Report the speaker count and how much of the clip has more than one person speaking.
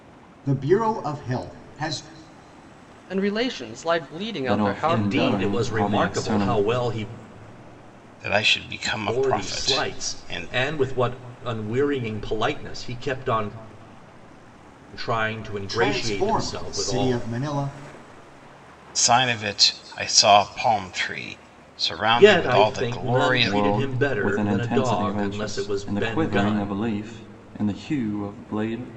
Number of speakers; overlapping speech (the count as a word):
five, about 34%